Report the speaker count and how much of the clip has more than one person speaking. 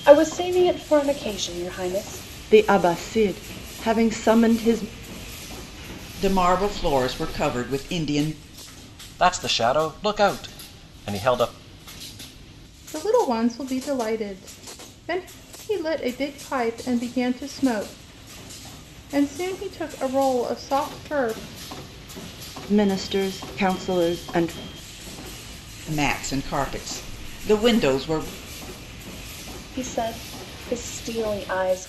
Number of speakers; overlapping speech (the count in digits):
5, no overlap